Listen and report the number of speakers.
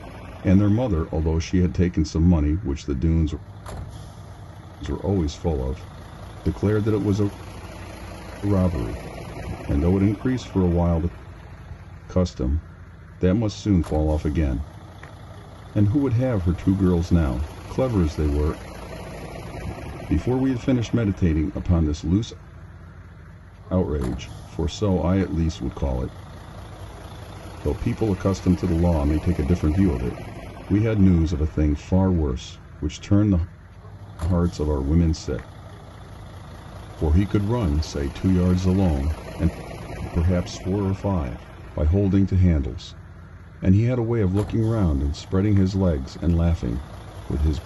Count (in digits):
1